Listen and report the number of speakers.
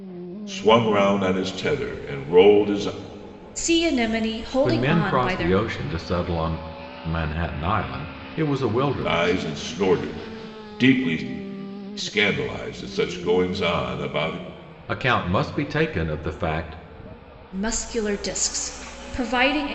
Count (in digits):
3